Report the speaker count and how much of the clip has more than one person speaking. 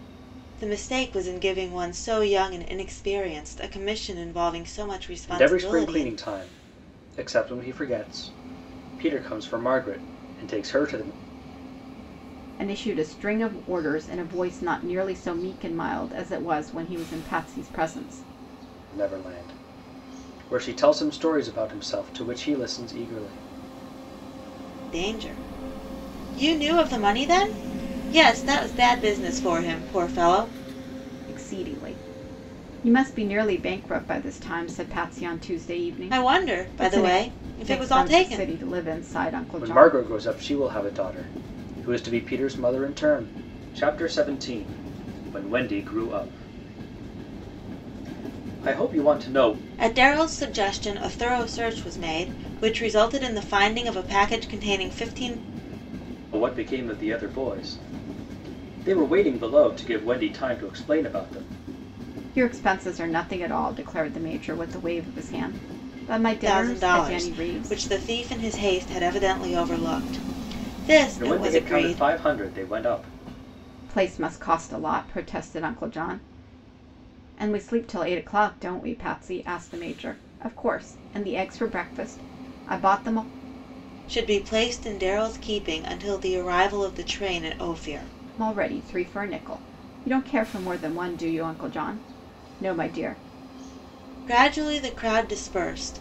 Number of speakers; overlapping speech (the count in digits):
3, about 6%